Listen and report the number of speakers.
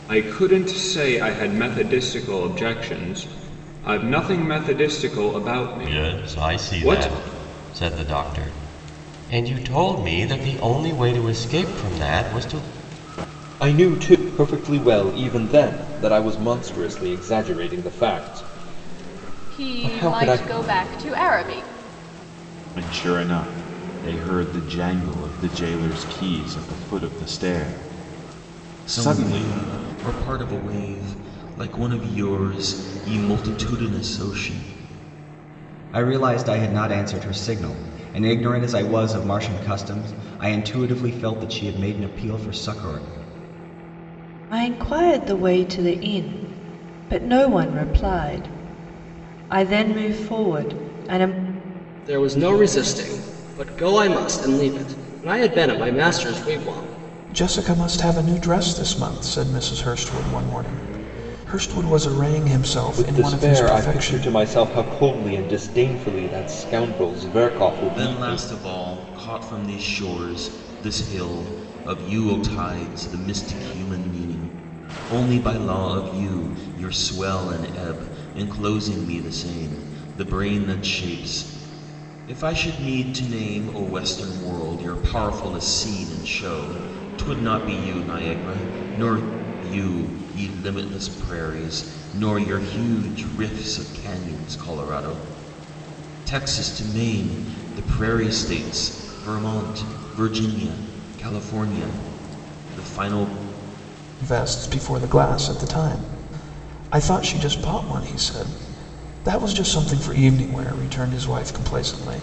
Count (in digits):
10